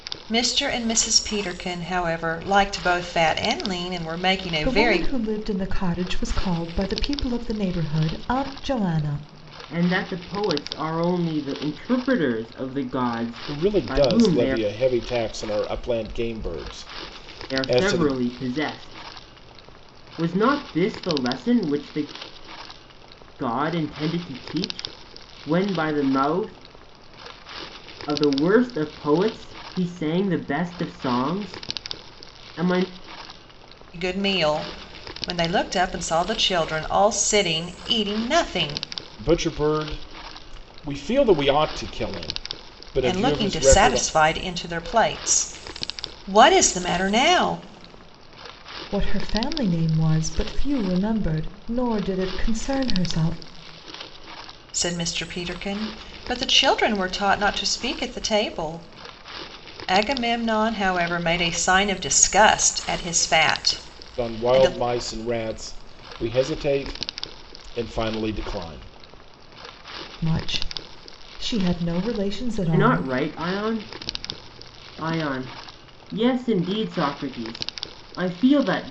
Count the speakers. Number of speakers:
4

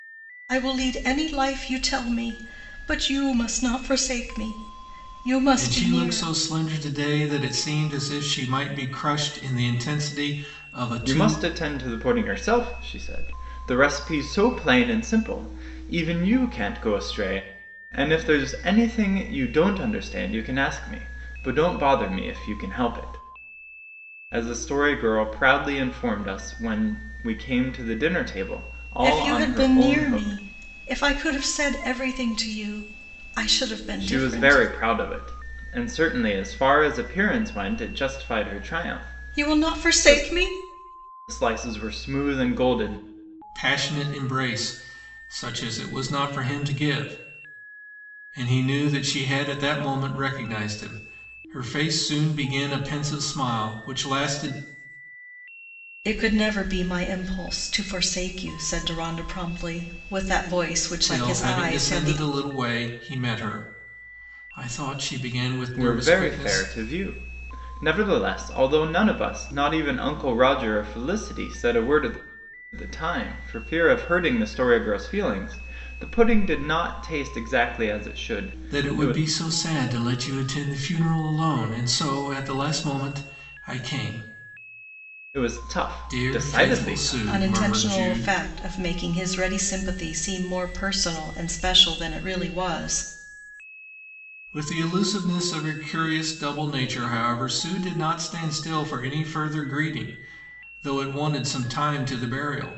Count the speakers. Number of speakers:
3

